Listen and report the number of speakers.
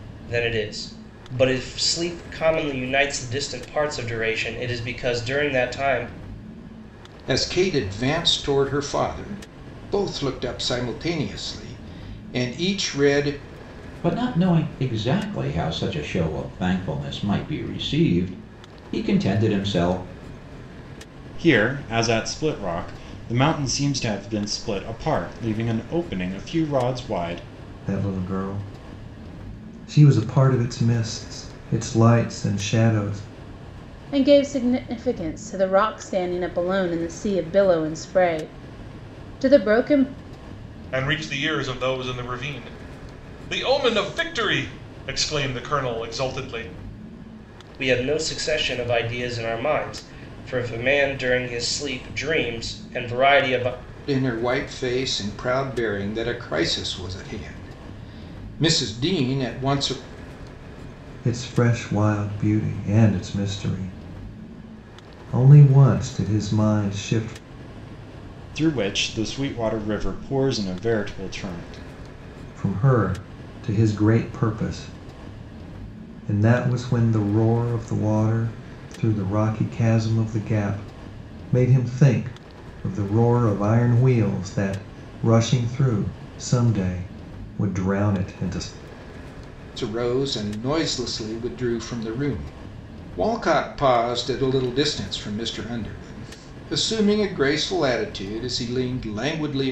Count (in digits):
7